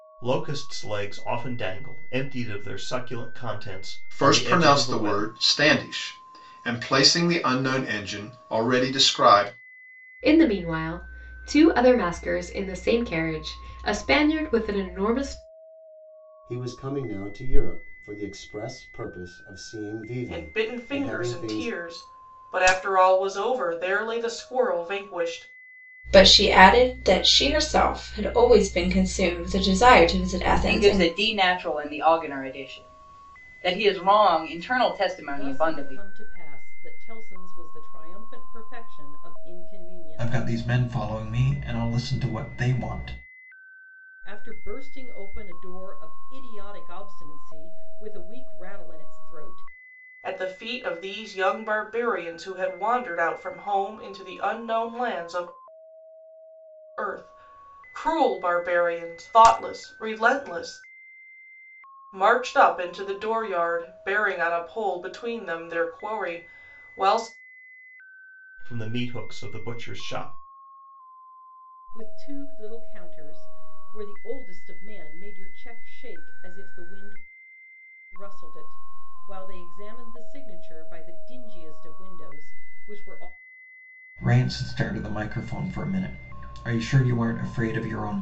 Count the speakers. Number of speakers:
9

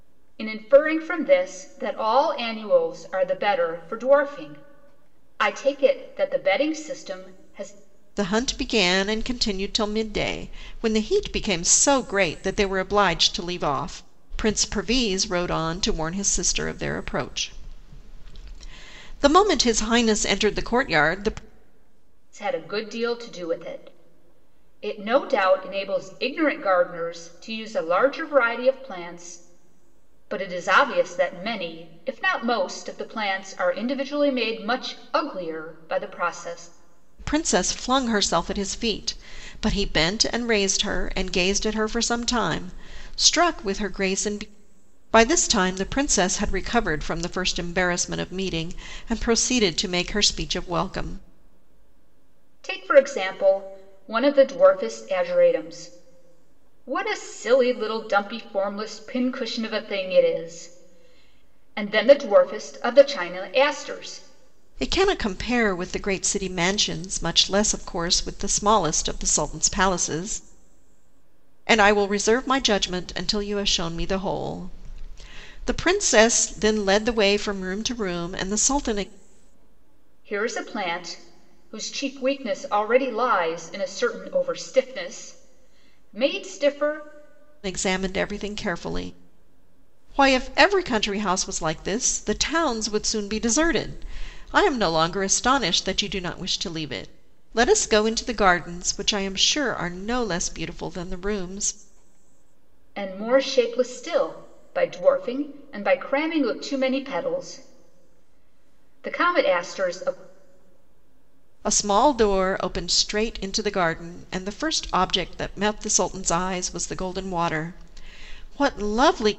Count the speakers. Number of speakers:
2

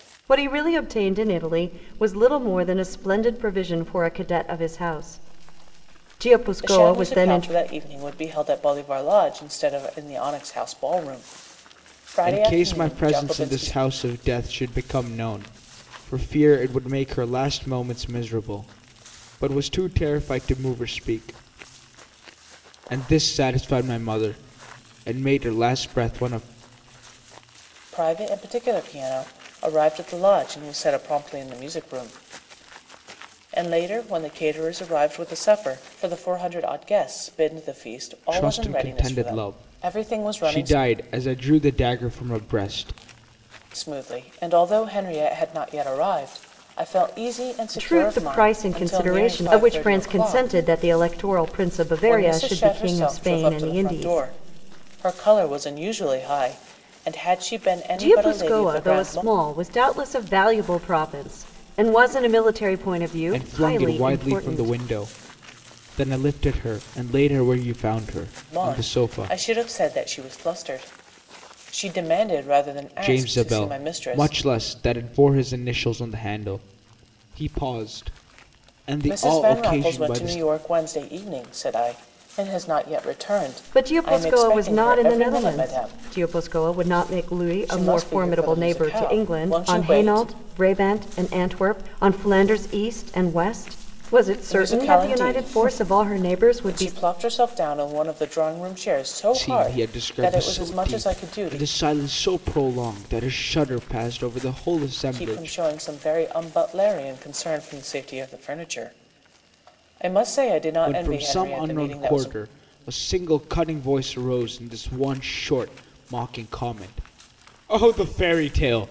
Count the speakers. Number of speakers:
3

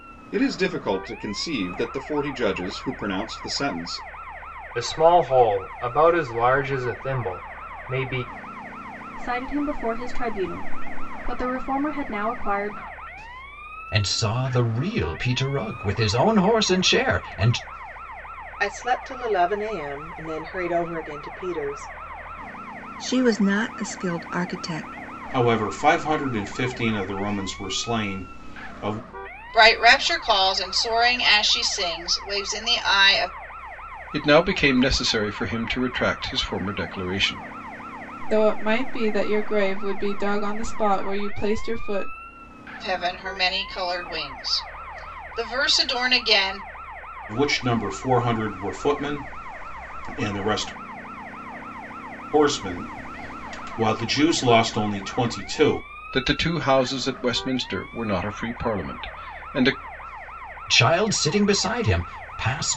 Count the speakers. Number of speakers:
10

